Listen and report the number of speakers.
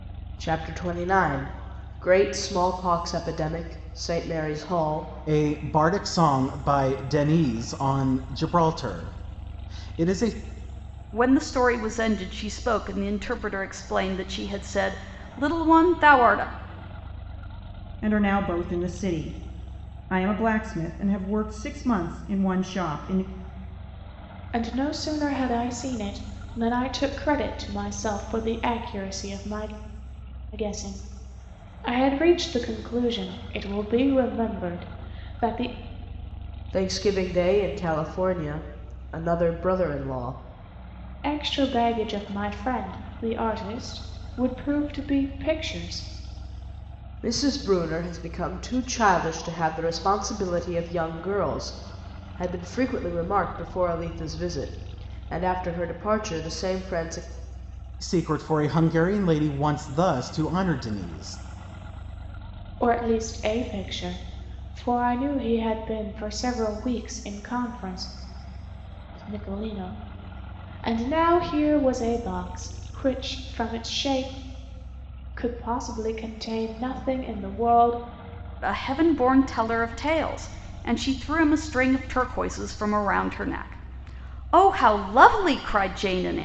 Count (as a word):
five